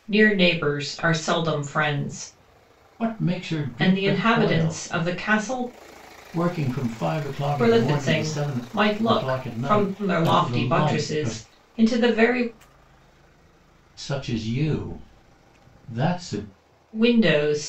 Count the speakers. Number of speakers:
2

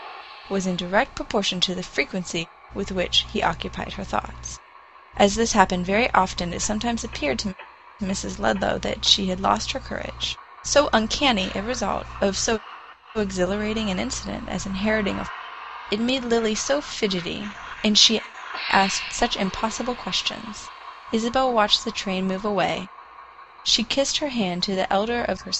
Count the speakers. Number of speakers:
1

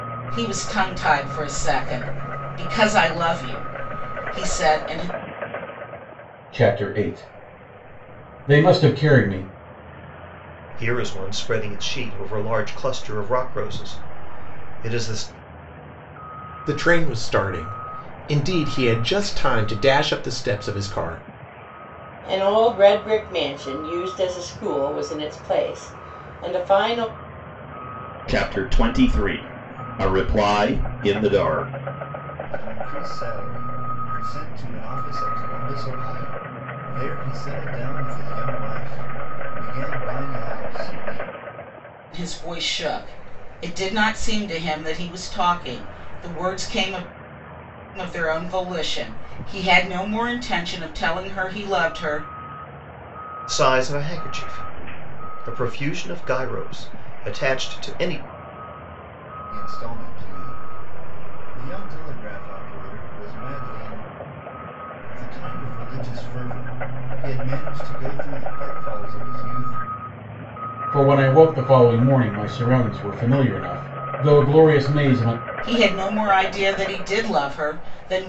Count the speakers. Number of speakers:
7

